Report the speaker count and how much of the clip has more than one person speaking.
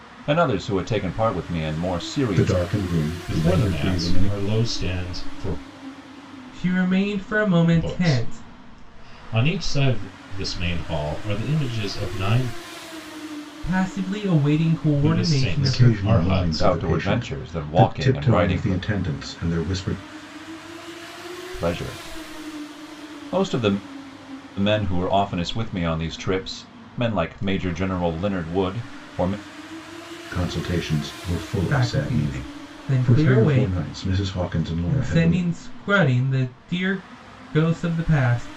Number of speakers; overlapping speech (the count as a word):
four, about 22%